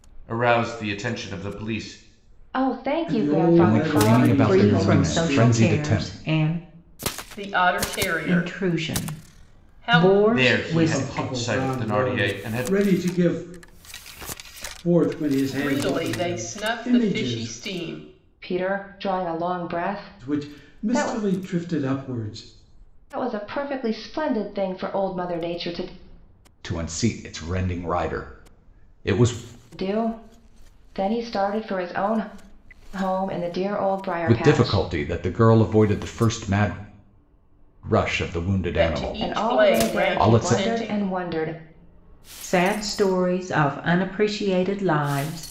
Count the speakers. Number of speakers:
six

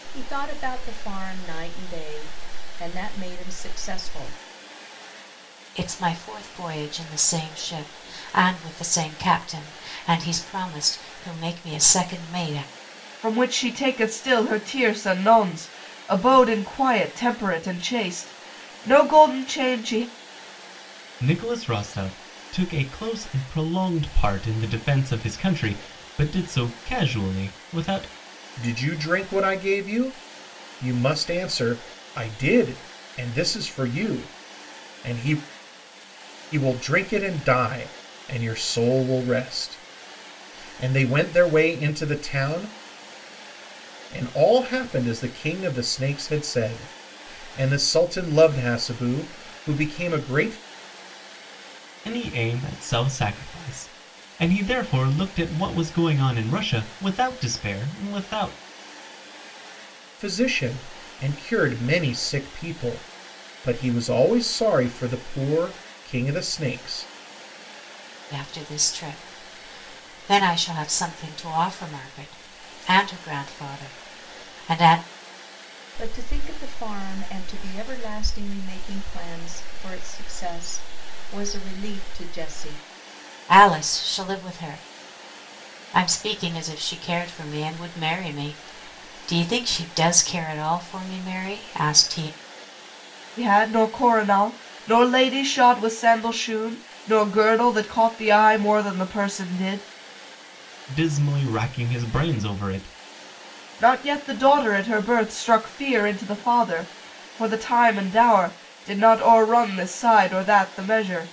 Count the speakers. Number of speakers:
five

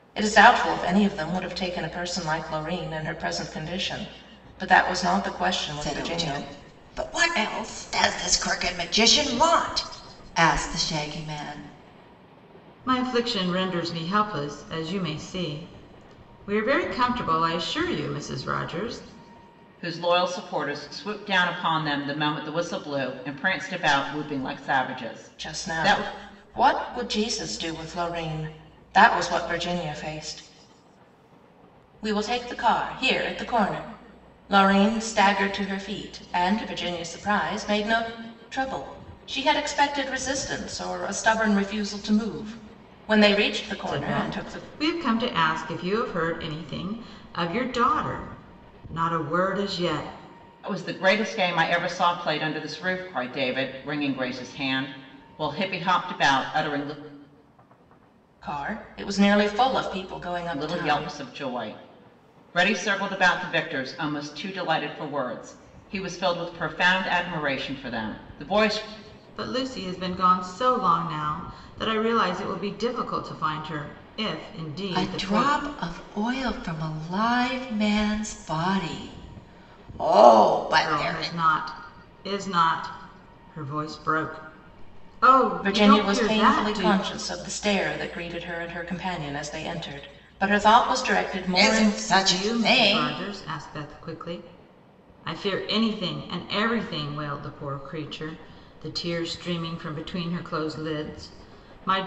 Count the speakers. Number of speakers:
four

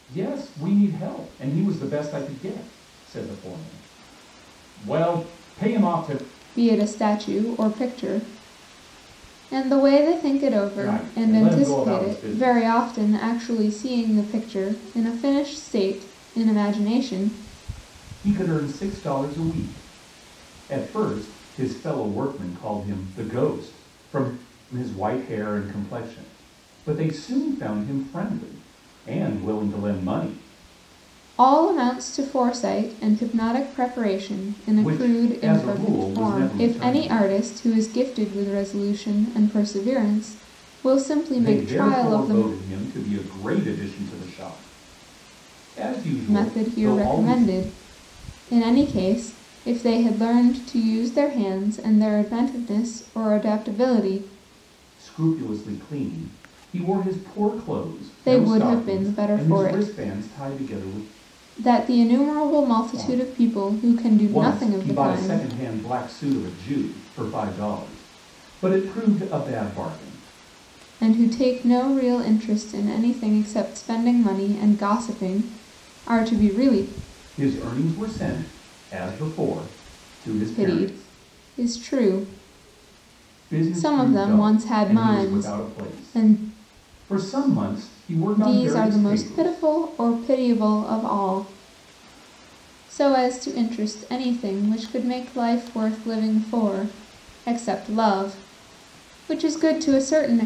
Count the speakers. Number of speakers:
two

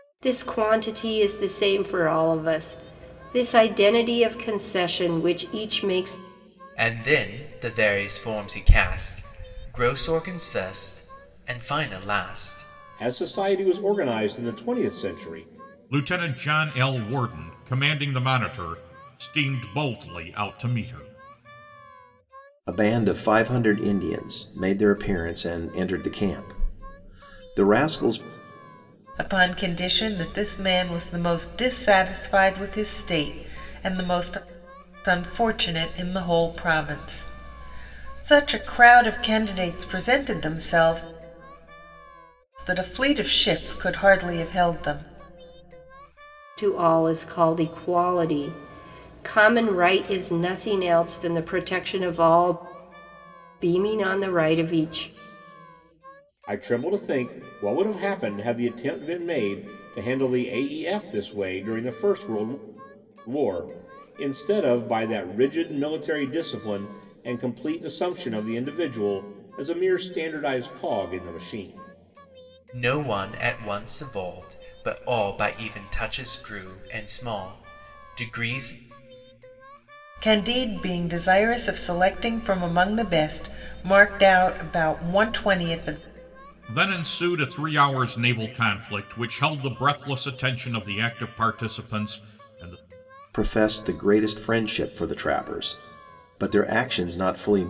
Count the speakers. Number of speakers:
six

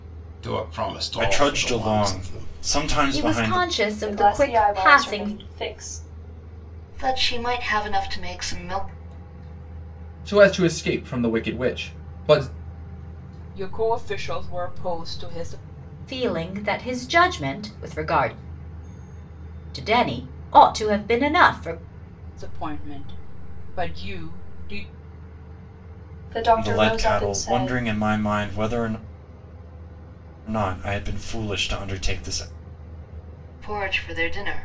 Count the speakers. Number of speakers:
seven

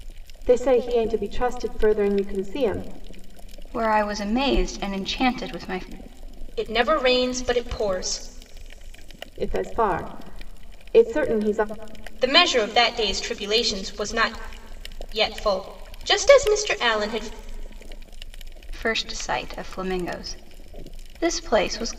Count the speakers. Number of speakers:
three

